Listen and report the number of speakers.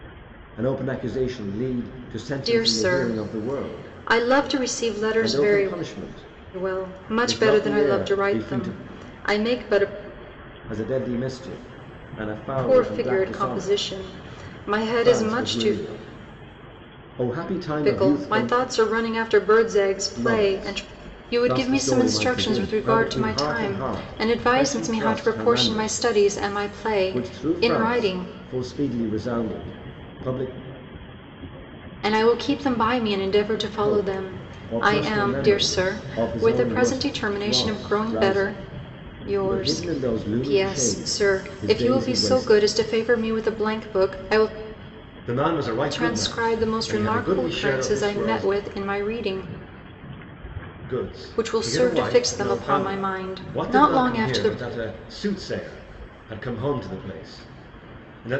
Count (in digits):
2